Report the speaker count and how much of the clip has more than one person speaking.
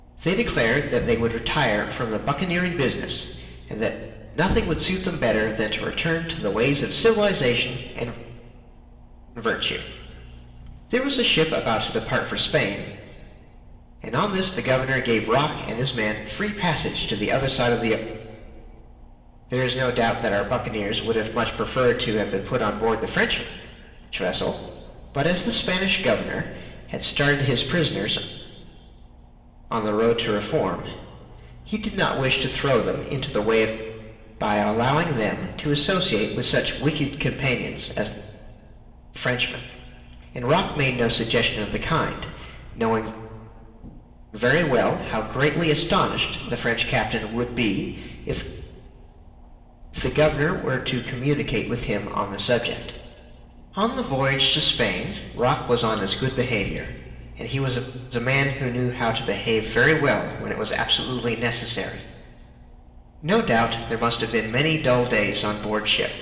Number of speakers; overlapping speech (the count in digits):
1, no overlap